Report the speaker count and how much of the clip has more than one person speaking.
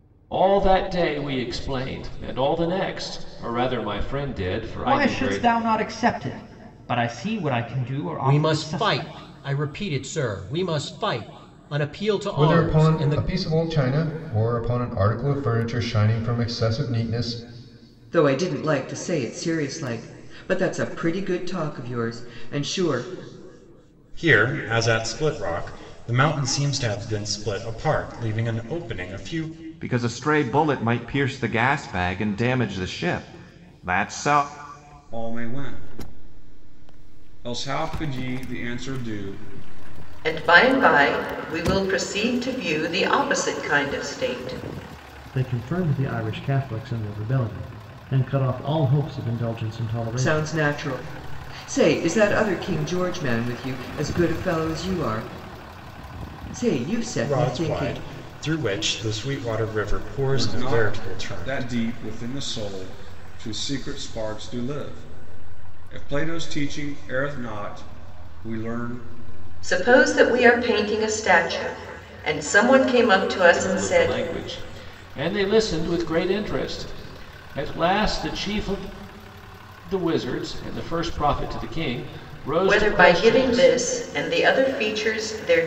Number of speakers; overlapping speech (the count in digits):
10, about 8%